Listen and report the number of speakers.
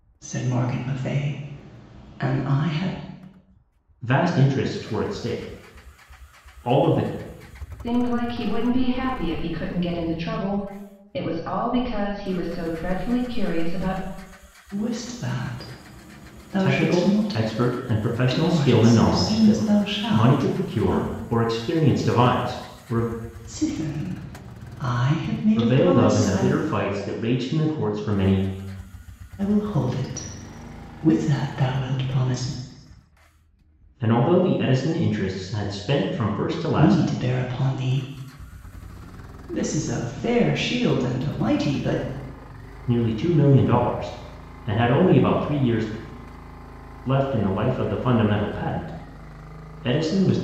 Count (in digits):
3